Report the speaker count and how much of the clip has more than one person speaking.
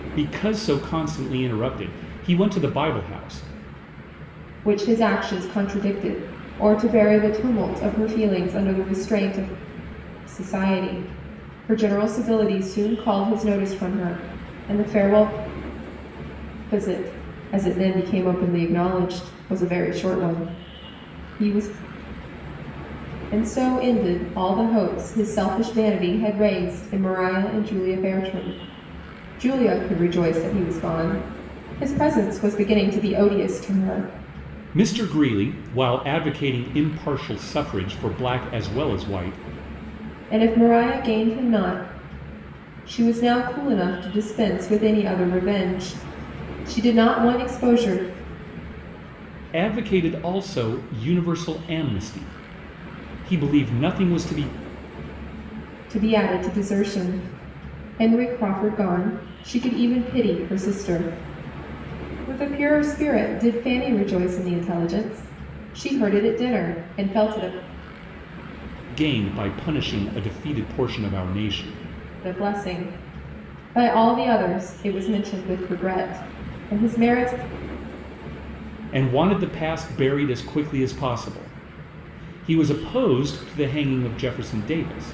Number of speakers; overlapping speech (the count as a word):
two, no overlap